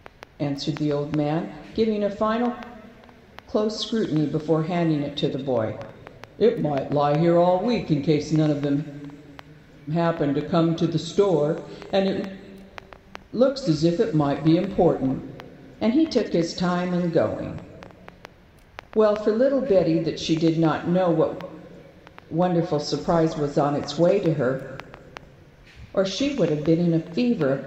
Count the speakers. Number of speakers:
1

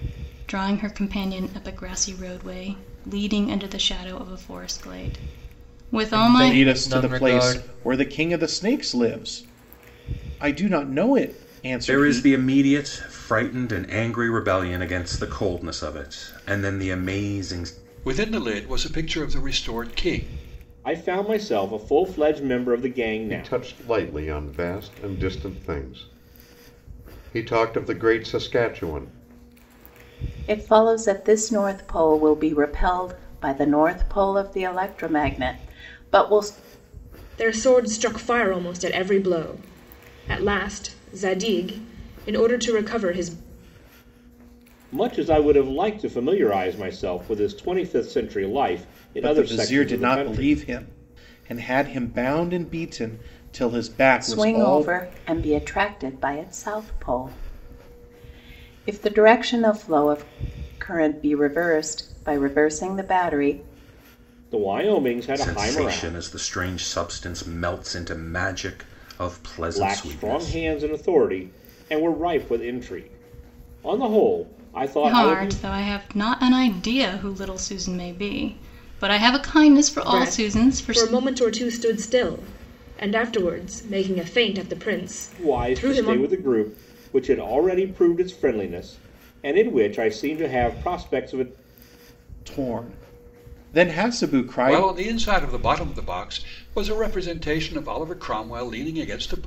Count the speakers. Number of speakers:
9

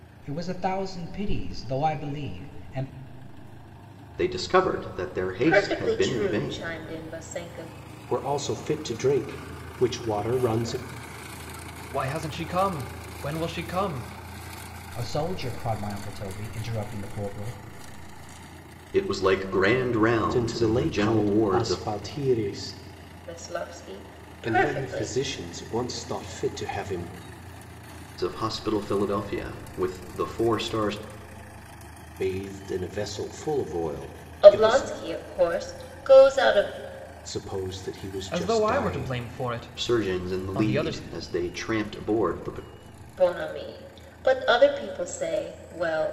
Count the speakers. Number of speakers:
5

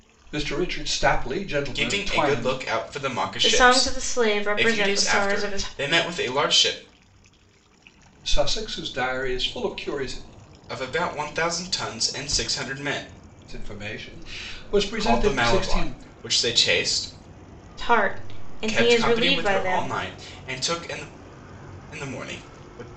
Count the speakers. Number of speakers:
3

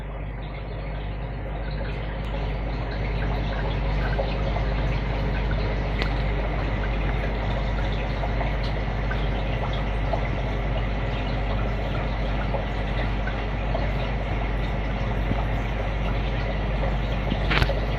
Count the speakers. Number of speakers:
0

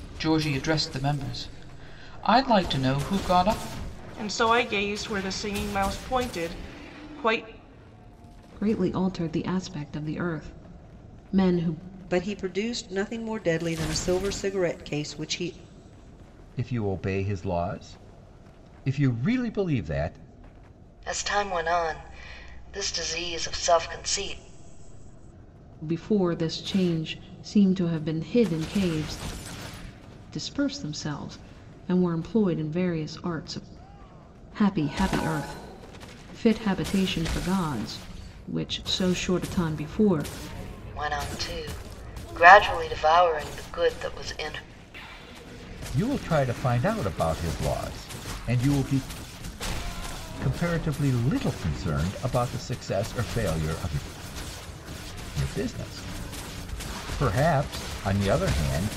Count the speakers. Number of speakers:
6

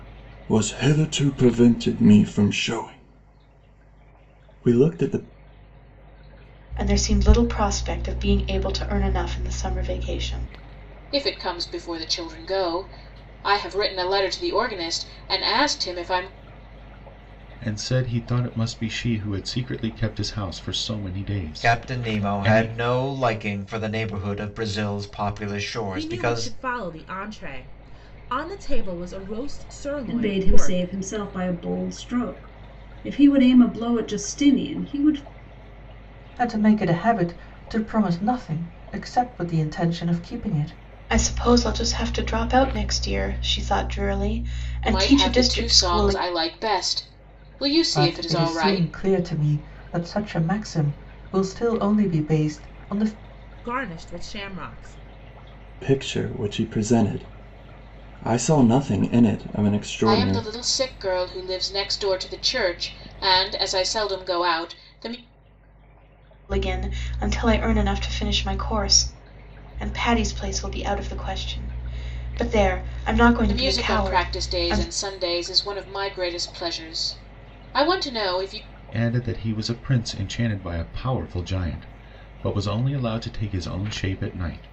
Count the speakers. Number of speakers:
8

